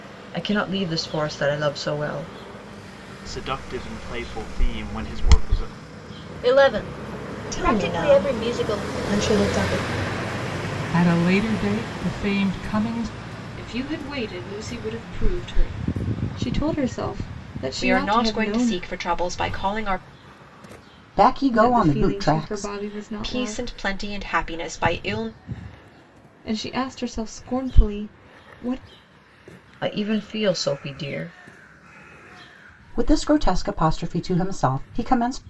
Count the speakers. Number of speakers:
9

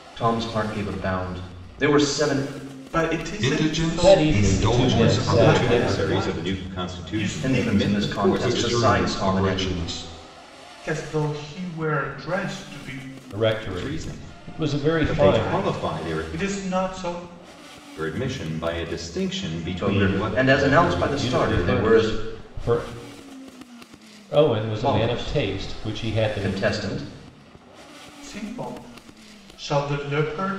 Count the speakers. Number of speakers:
5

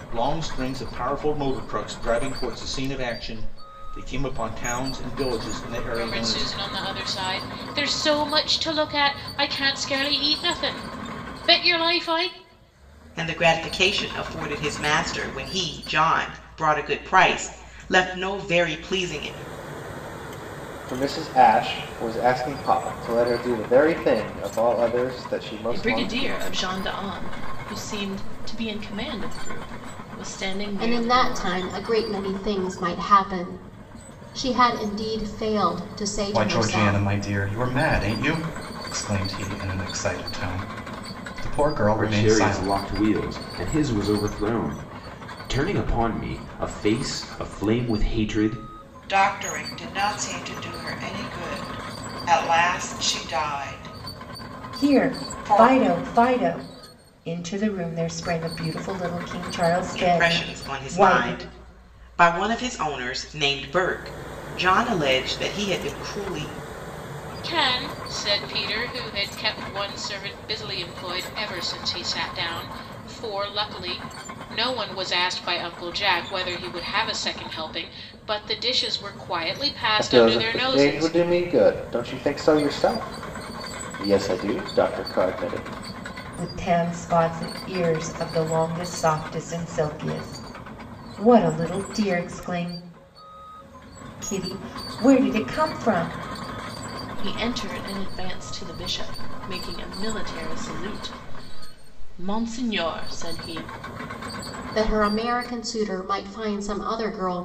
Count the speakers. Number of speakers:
10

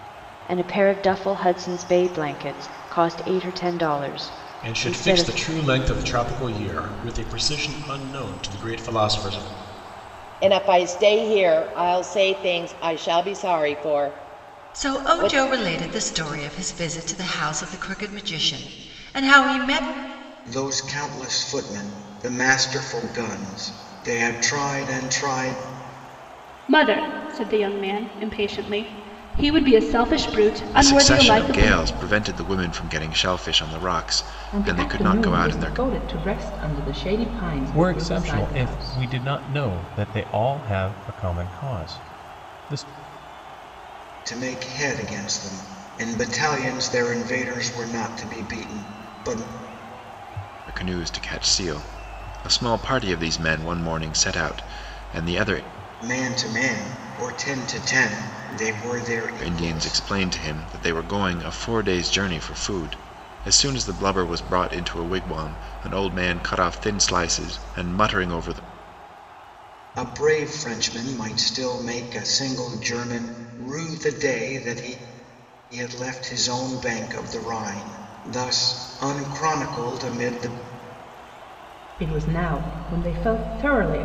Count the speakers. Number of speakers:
9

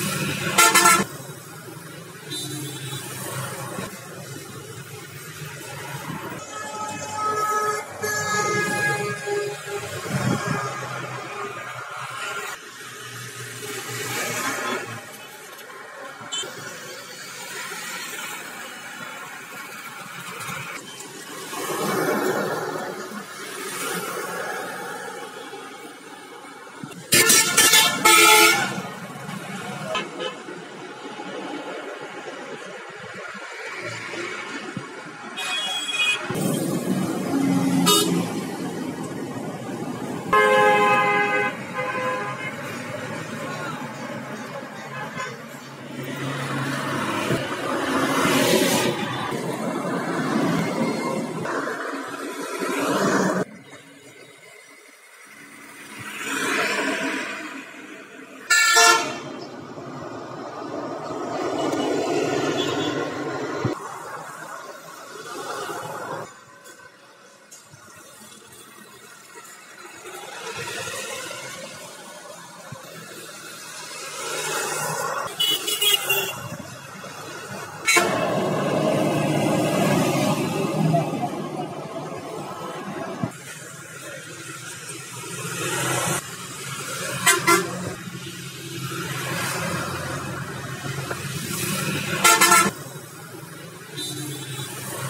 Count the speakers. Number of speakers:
0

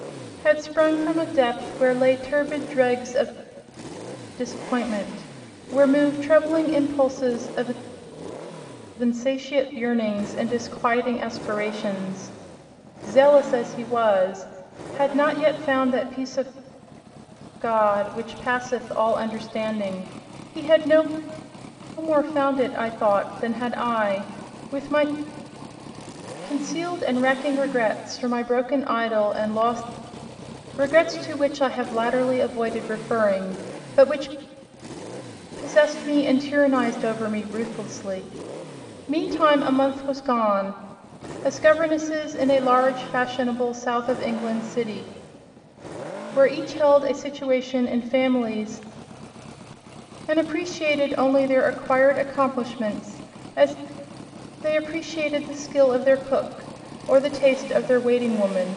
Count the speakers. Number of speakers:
1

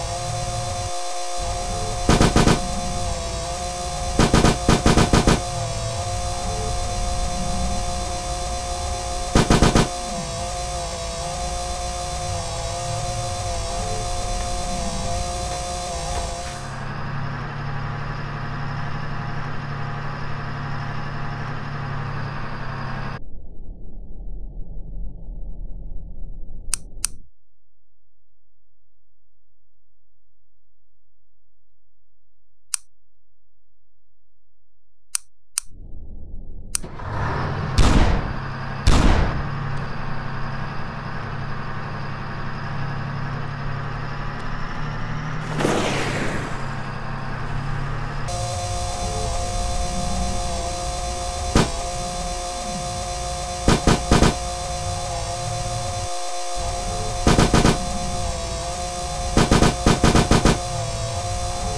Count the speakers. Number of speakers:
0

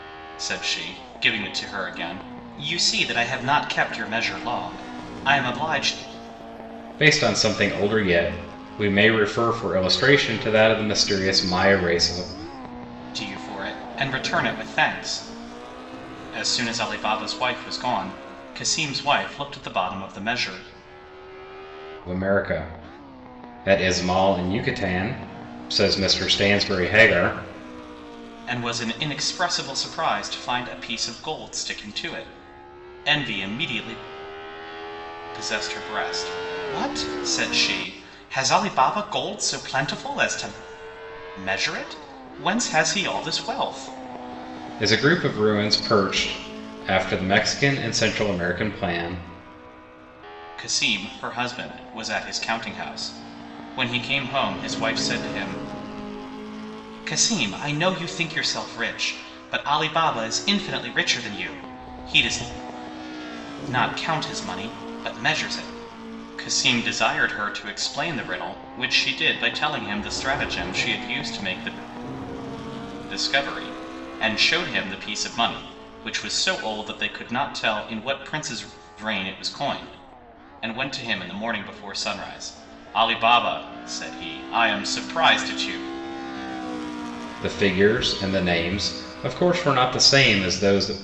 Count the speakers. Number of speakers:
2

